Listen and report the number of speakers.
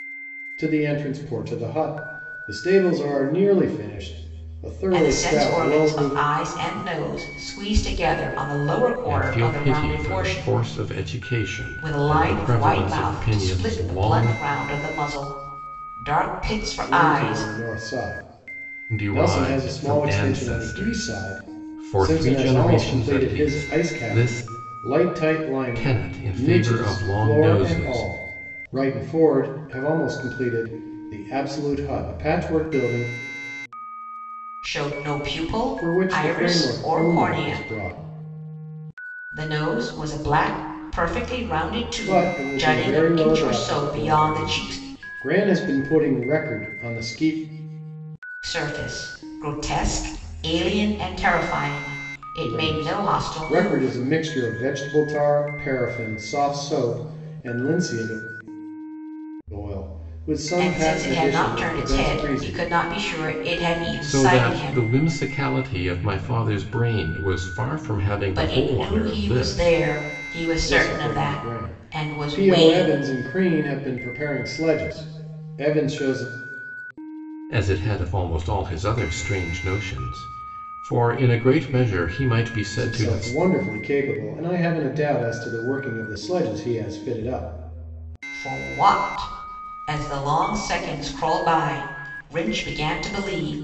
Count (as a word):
three